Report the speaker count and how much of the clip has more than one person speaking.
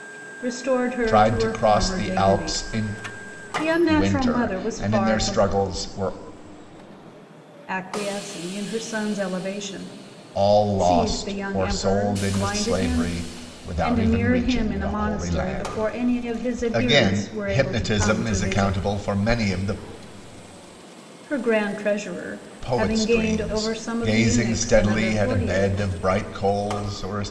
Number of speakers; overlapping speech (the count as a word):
two, about 49%